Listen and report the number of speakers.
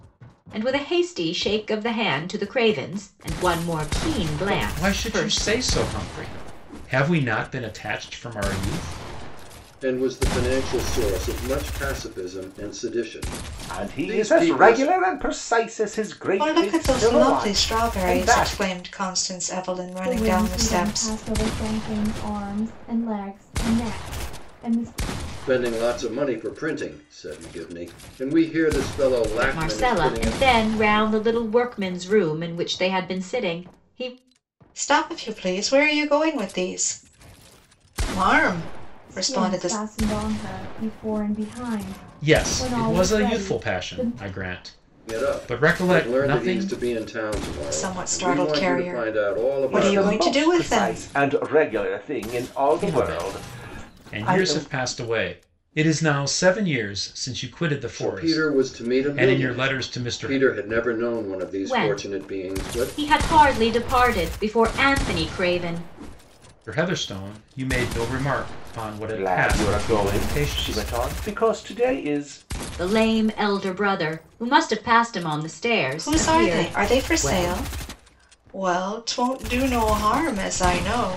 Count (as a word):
six